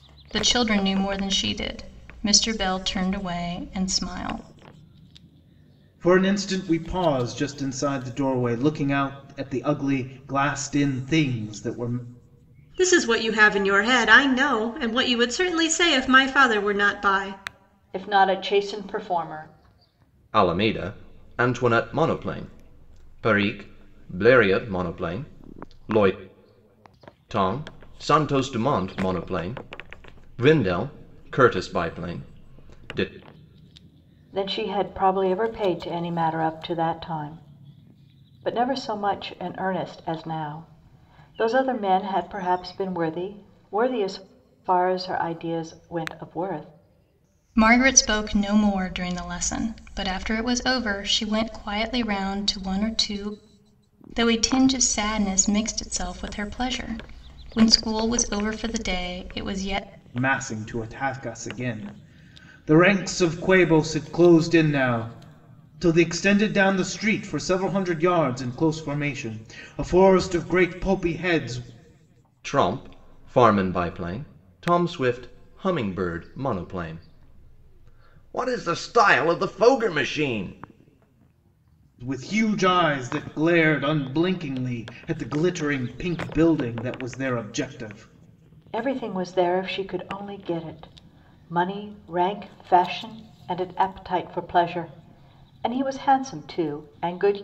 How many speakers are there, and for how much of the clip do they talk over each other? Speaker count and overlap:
5, no overlap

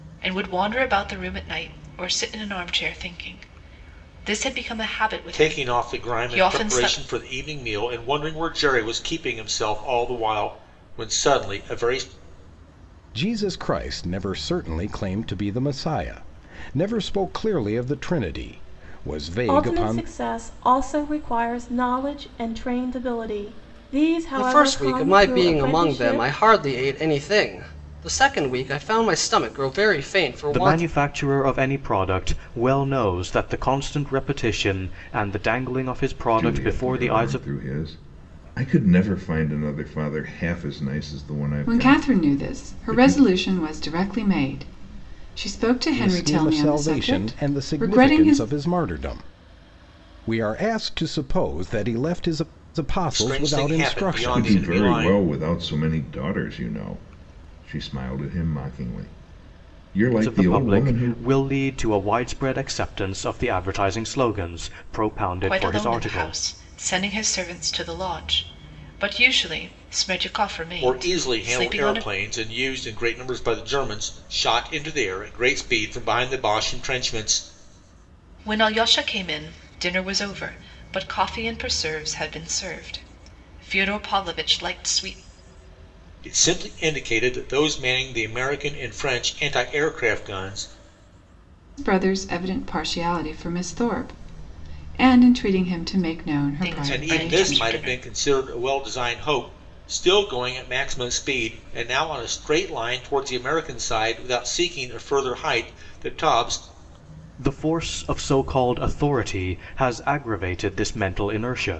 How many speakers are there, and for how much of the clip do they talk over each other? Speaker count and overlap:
8, about 15%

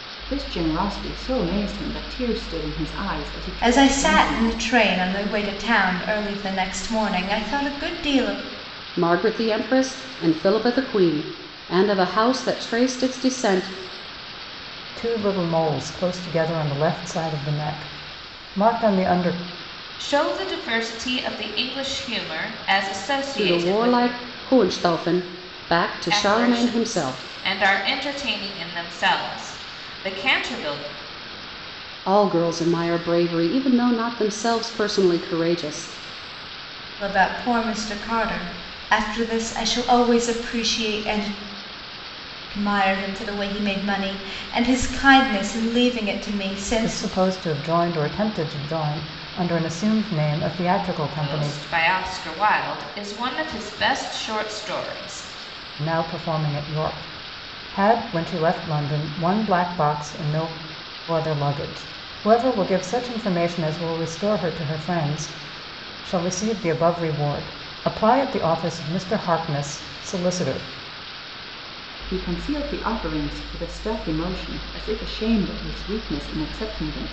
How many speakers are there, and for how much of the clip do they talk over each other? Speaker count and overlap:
5, about 5%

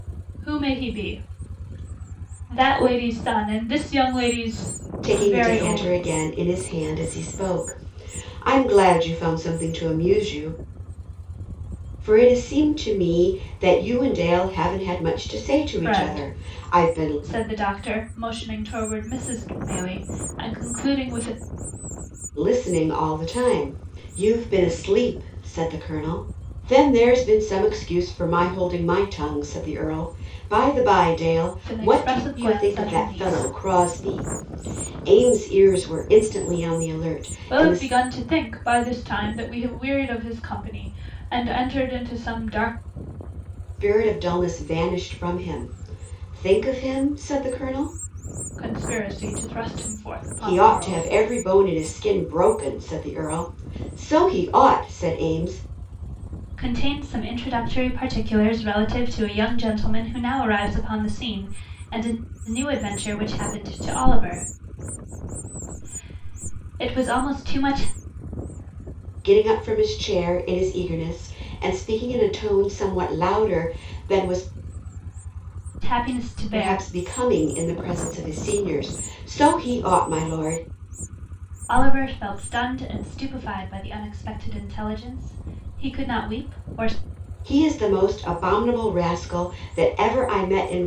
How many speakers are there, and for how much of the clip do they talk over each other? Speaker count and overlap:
2, about 6%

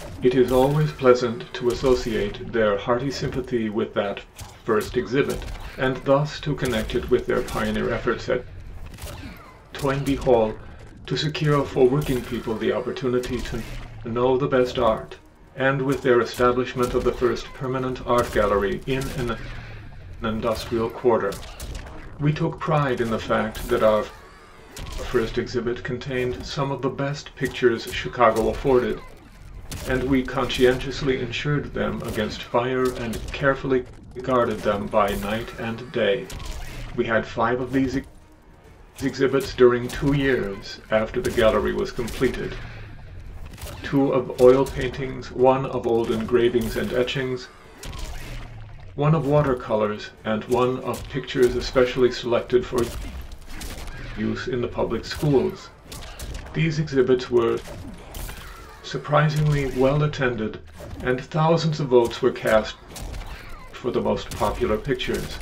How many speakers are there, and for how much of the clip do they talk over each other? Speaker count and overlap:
1, no overlap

